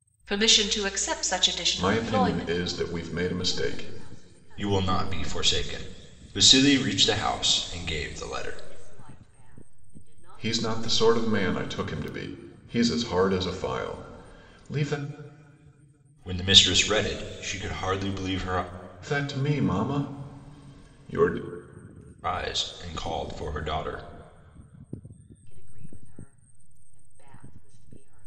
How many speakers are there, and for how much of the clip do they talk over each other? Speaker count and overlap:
4, about 9%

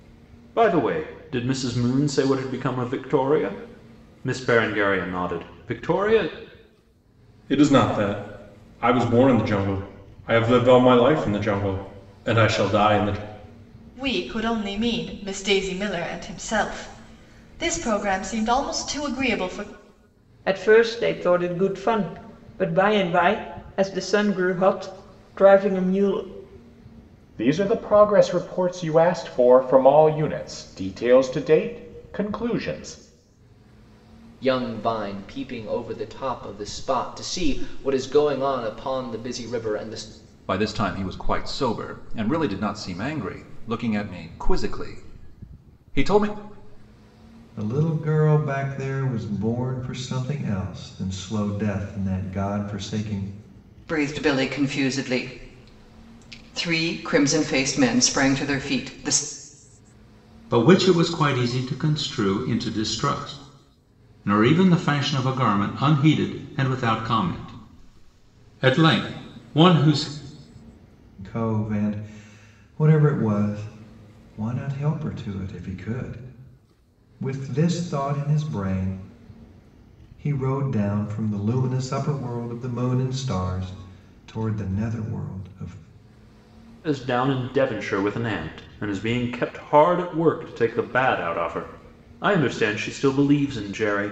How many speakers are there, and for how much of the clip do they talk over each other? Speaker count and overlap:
10, no overlap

